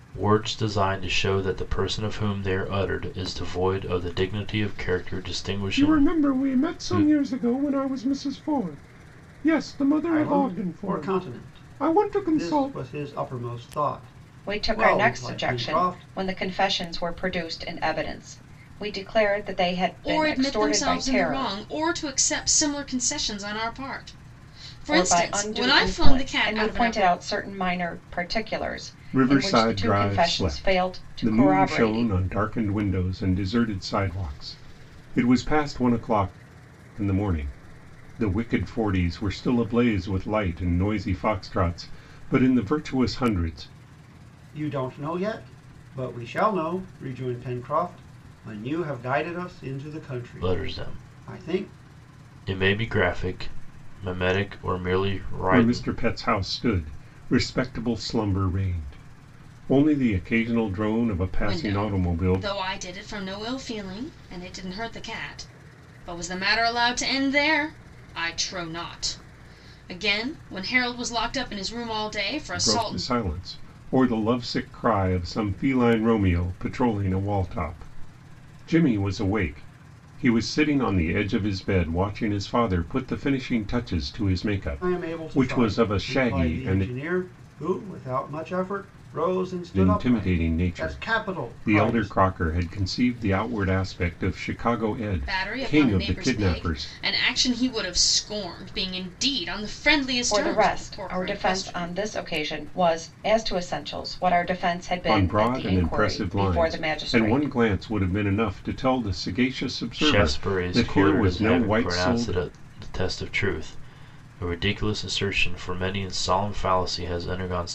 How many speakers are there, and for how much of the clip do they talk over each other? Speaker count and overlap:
five, about 25%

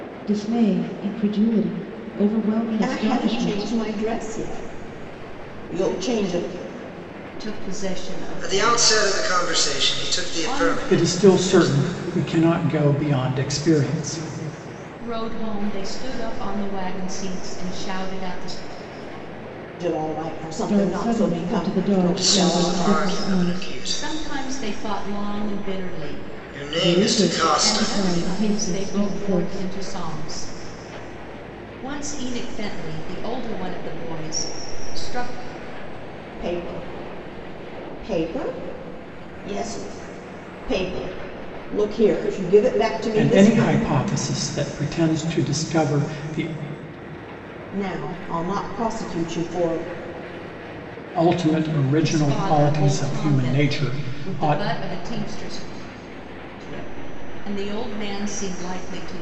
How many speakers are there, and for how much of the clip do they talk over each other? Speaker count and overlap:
five, about 24%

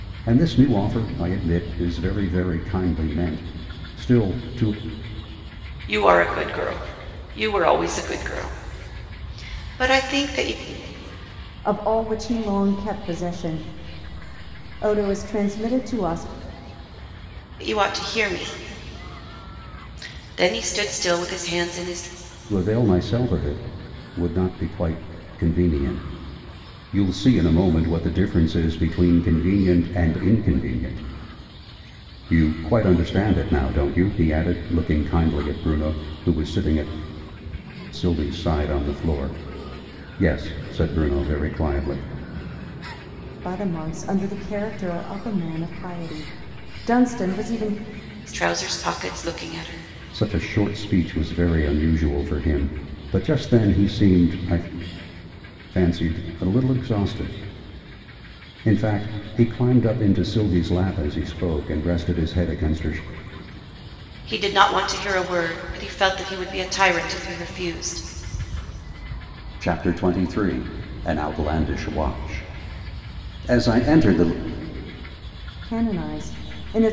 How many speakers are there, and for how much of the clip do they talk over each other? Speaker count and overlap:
three, no overlap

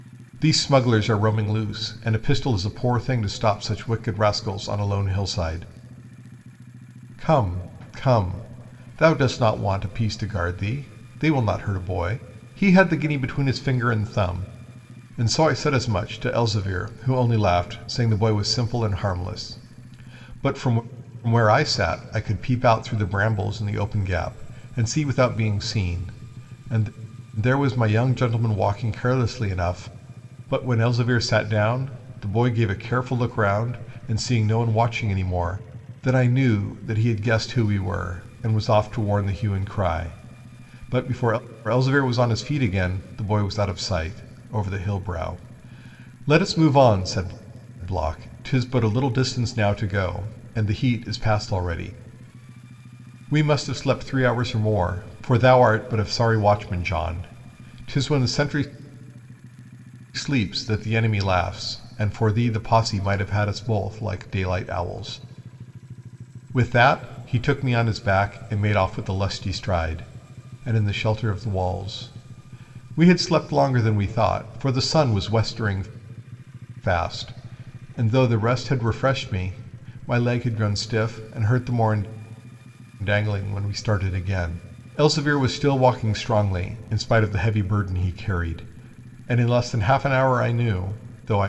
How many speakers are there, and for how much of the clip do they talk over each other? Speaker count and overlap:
one, no overlap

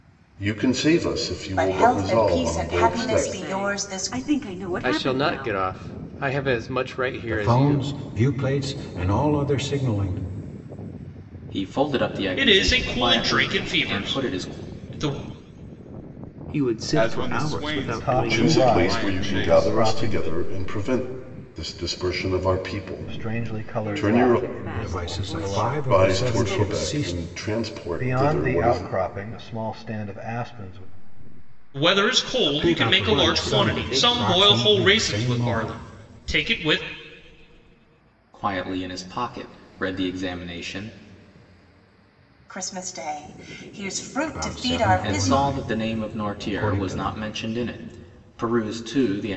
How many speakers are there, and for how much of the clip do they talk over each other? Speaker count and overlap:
ten, about 43%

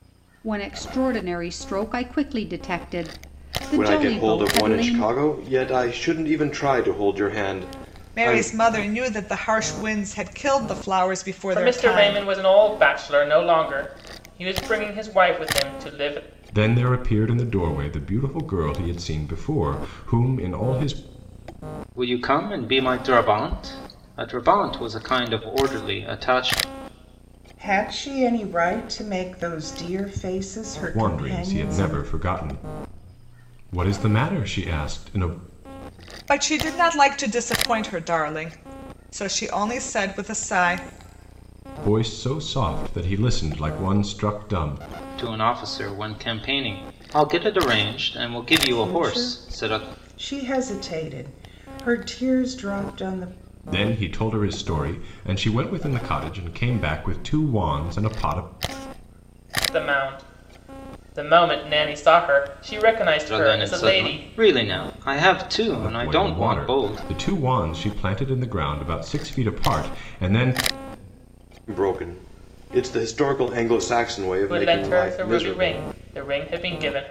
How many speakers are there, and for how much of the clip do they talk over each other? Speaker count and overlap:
seven, about 11%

